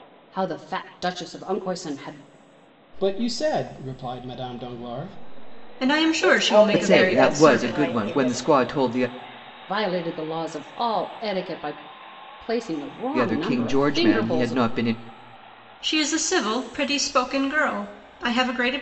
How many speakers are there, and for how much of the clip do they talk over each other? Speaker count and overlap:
5, about 20%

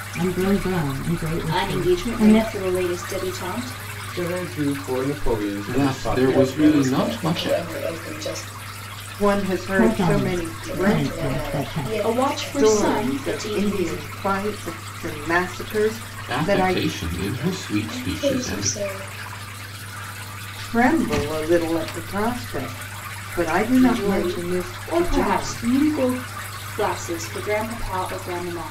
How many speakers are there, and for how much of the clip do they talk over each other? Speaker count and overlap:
6, about 39%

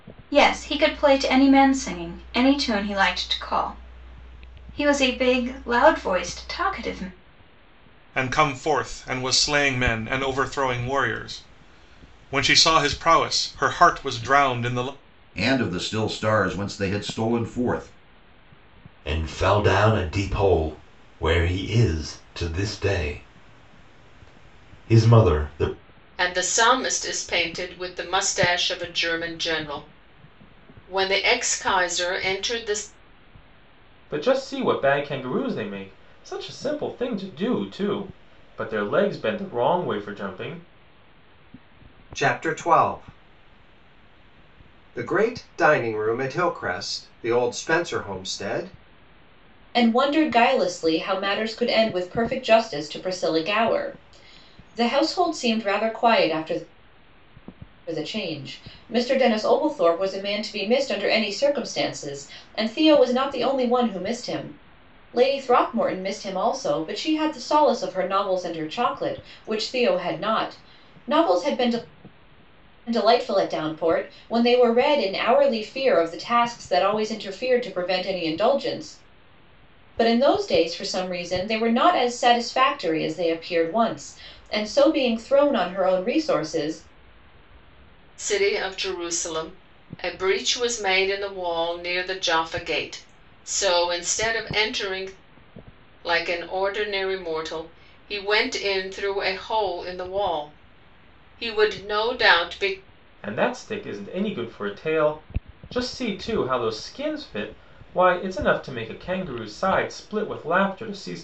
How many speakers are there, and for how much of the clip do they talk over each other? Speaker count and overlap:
8, no overlap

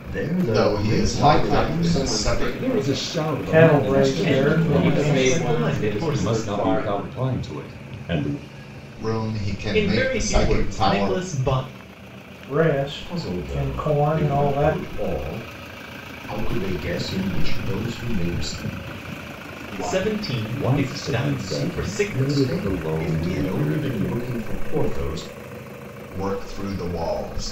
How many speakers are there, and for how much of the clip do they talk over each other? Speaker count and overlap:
7, about 51%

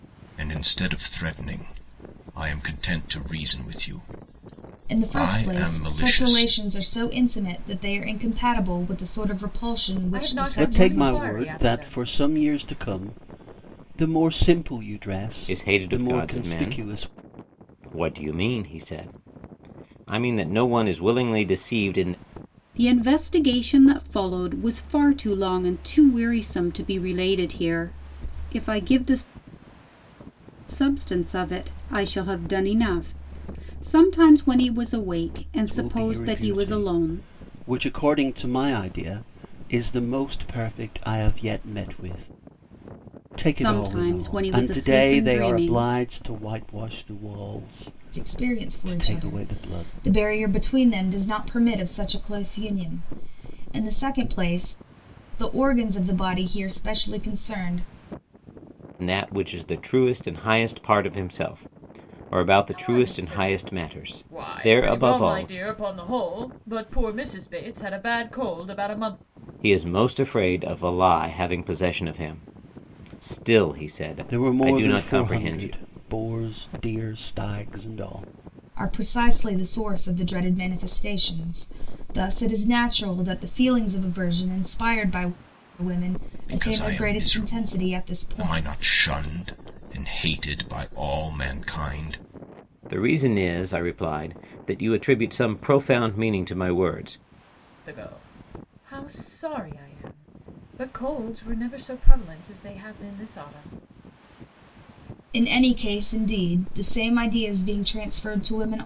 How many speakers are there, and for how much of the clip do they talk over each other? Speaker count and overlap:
6, about 16%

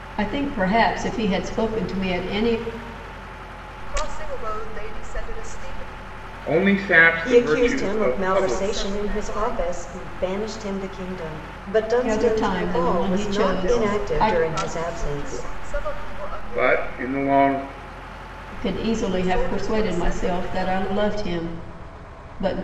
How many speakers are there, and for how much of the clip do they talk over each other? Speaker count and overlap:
4, about 44%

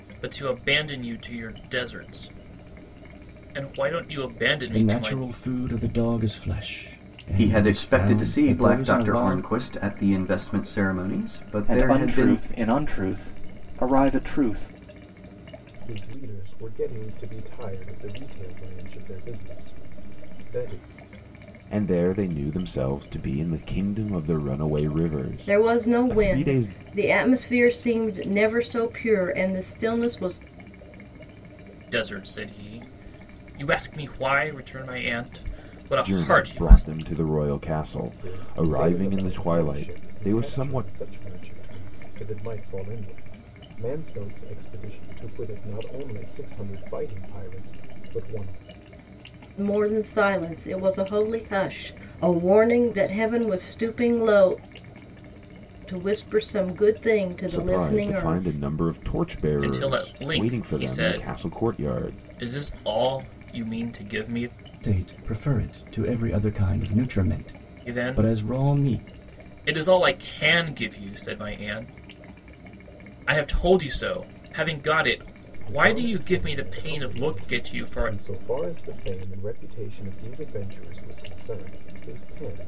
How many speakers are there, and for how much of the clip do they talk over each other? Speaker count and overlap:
7, about 20%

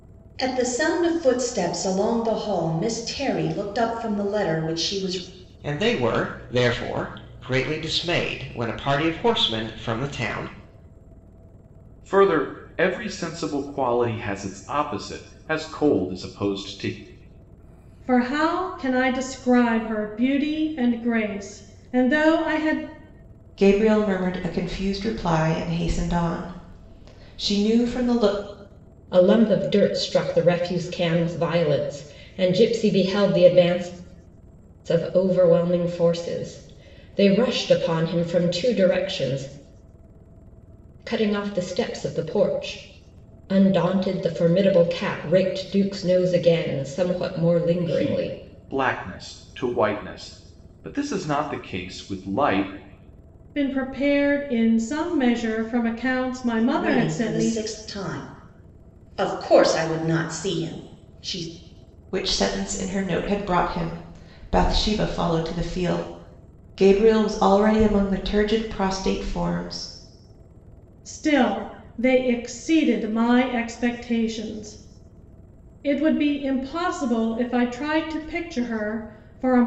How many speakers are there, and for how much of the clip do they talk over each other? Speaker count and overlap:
6, about 2%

